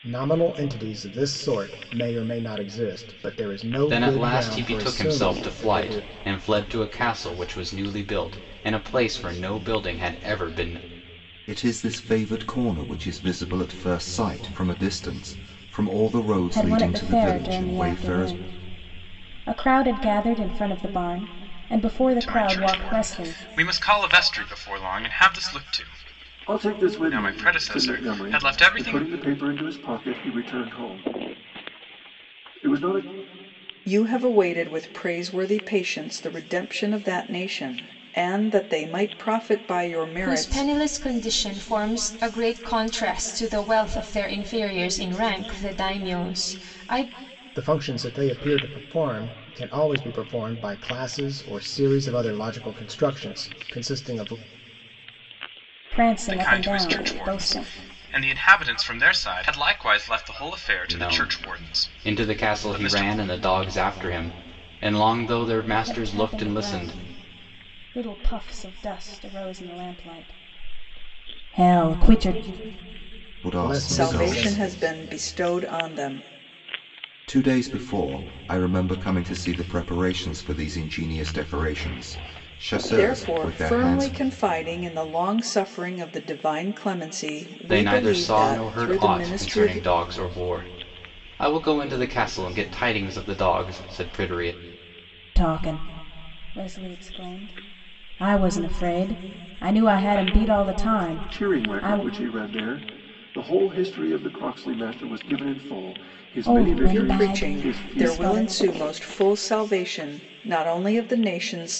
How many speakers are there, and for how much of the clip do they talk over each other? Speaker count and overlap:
8, about 19%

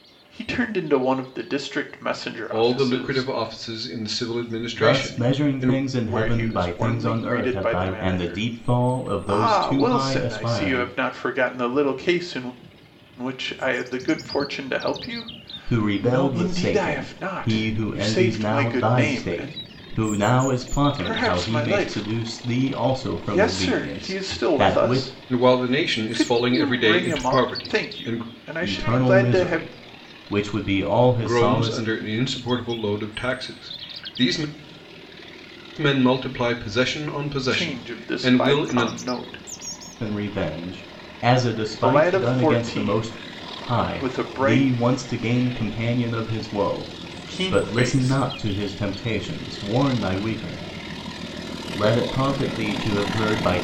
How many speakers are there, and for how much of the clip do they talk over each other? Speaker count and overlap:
3, about 42%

